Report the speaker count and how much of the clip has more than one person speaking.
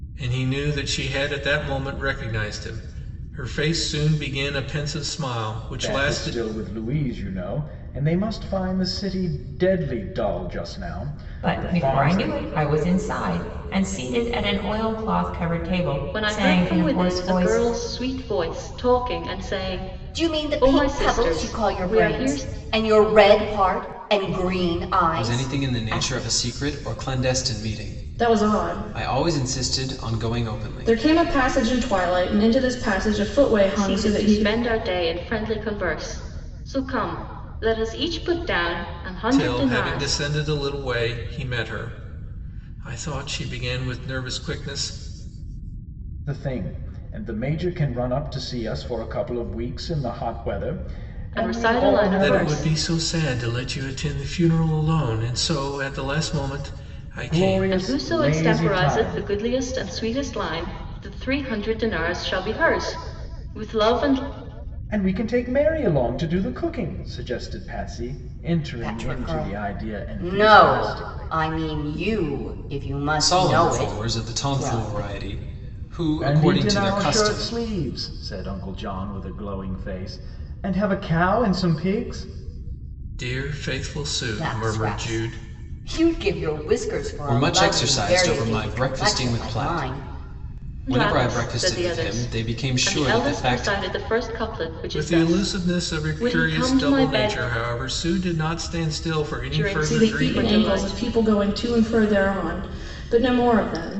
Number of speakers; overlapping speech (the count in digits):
7, about 31%